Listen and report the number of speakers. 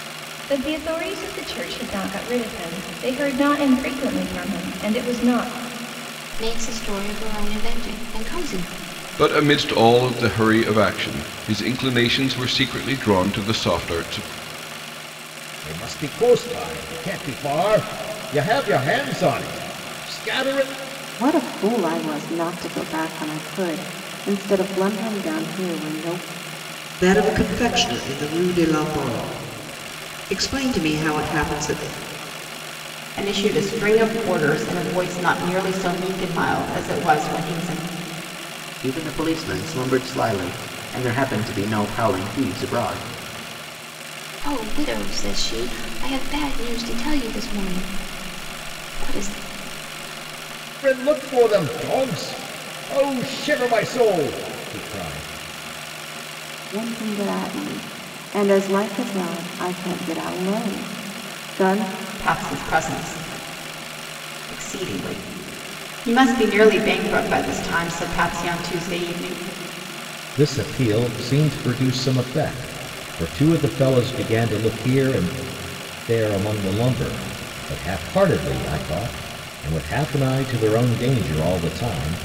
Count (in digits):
8